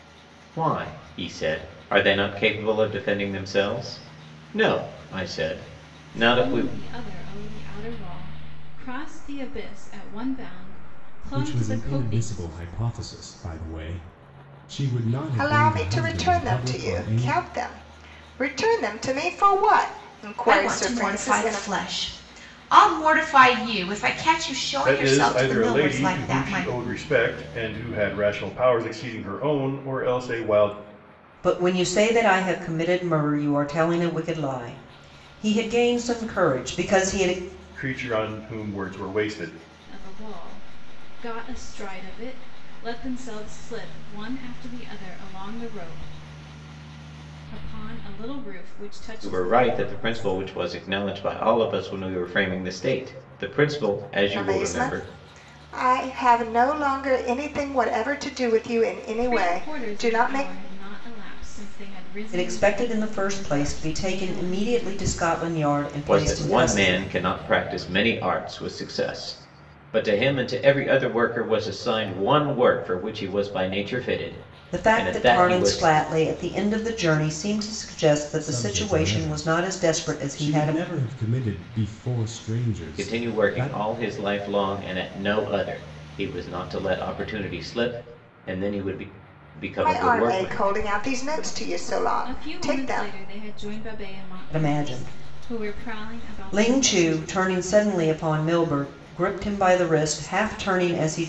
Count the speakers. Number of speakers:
7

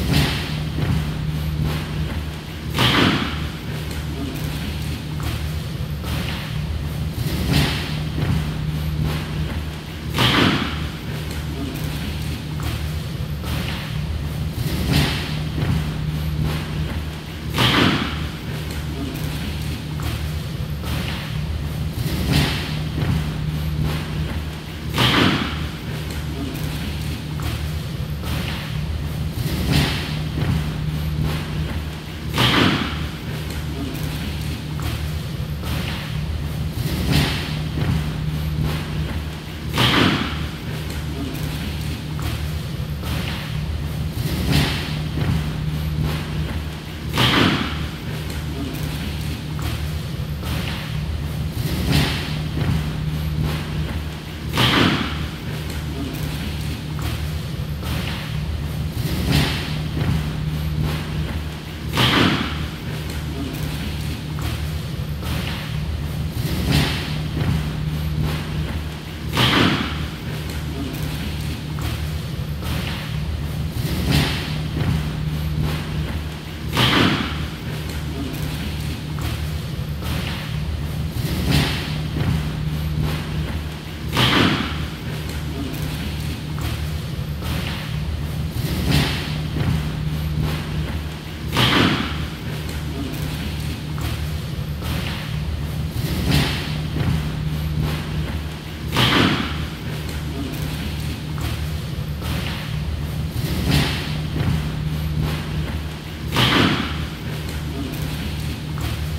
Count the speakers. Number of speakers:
0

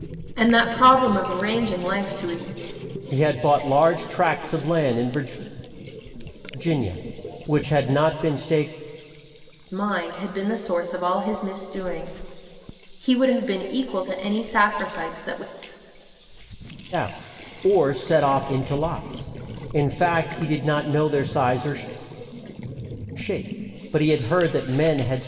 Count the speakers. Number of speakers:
2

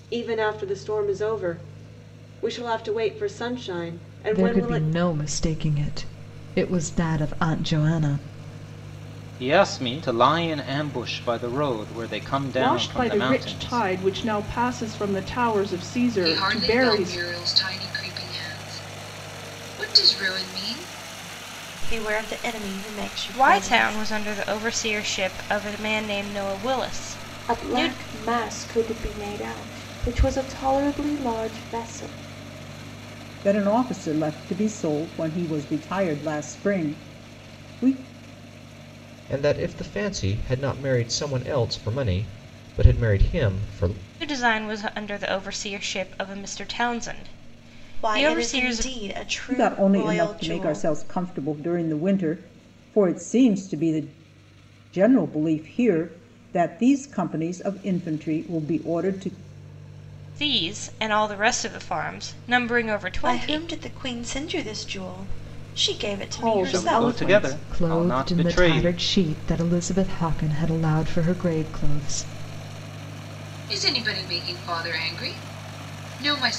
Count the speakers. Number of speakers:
10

